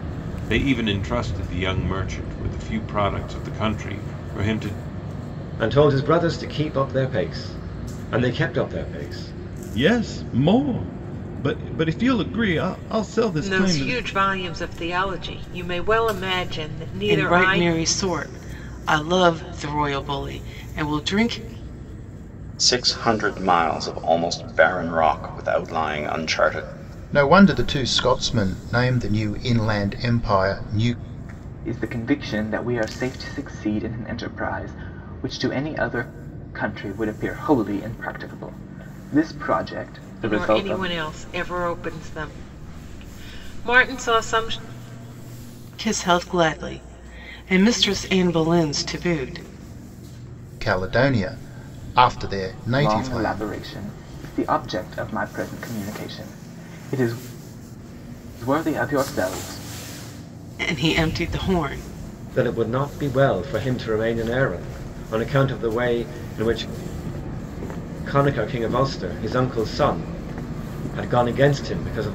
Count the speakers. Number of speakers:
eight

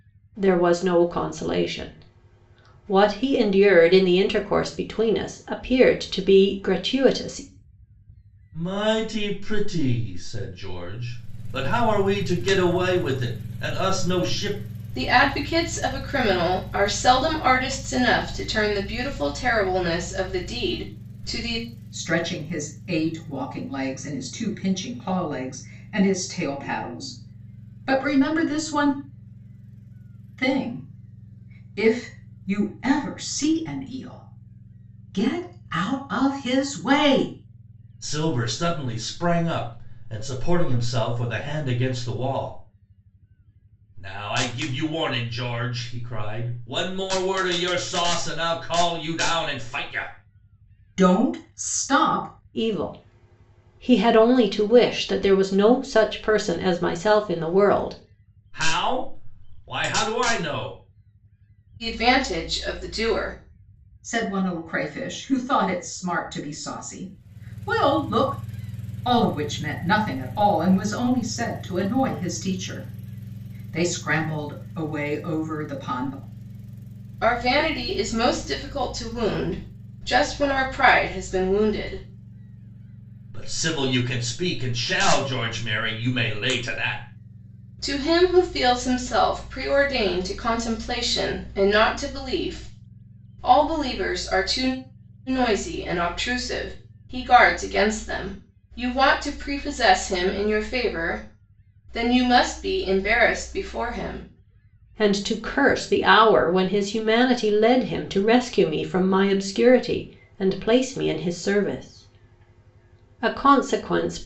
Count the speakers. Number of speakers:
four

